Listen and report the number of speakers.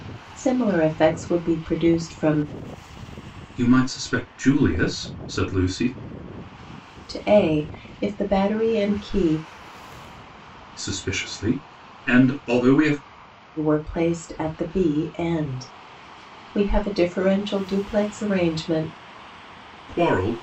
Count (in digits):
2